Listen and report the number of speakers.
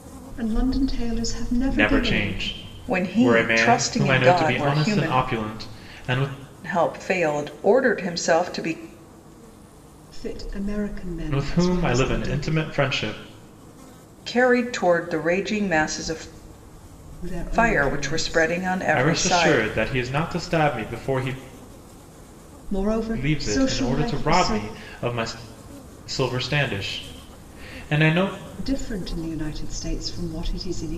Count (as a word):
three